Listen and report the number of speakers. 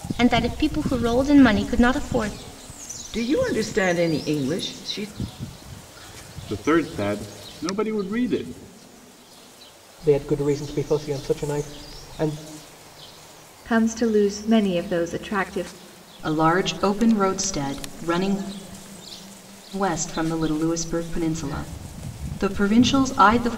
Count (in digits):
6